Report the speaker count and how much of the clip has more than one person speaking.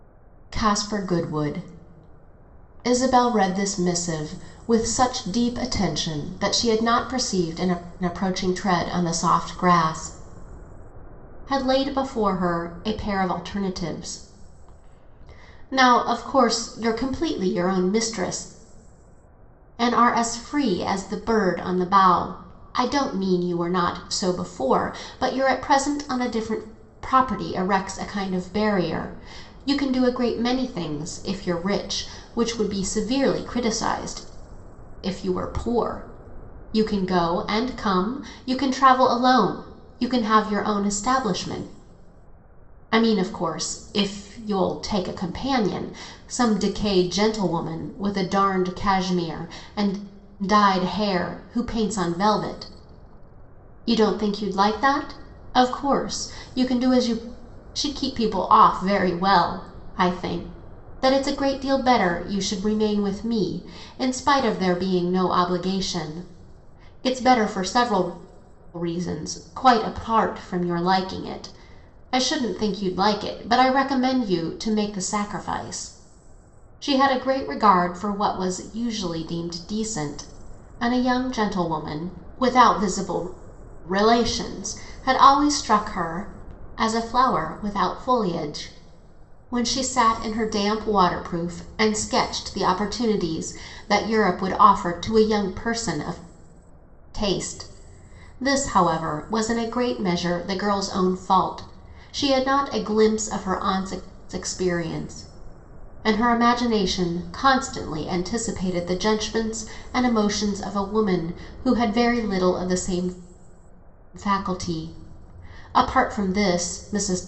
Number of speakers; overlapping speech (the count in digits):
1, no overlap